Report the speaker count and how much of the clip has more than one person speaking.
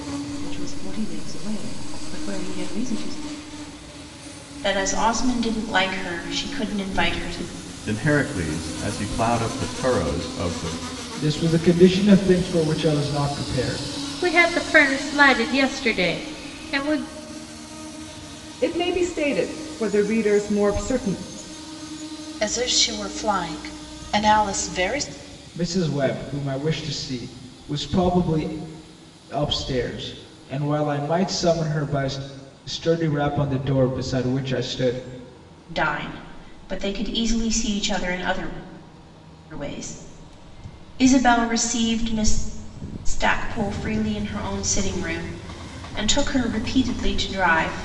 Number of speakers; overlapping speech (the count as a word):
seven, no overlap